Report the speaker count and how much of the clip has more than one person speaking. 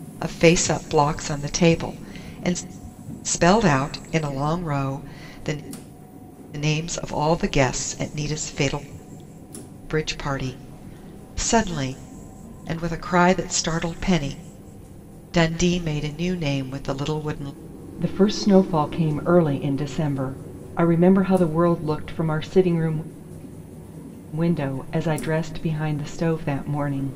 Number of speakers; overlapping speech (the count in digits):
1, no overlap